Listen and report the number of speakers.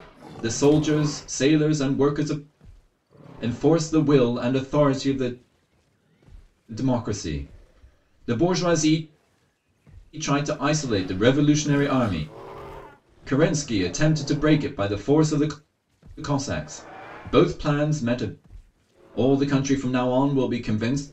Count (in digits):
1